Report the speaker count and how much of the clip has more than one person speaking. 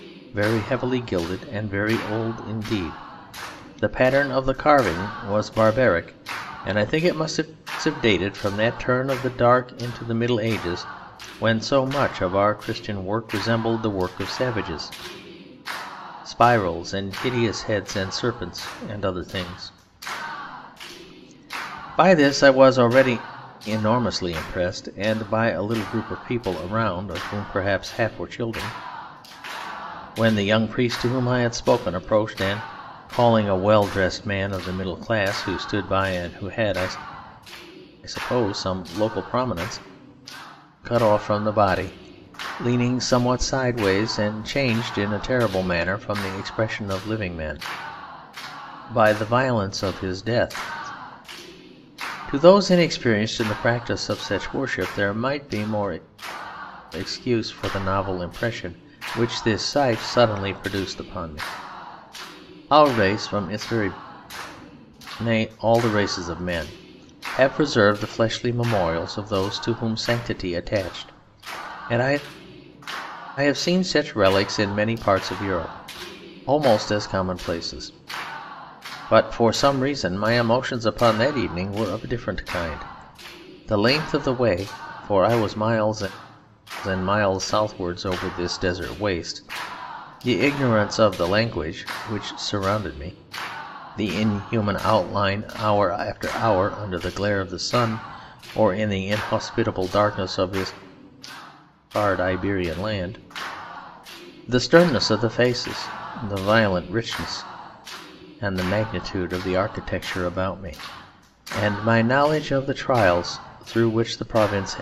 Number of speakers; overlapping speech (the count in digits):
1, no overlap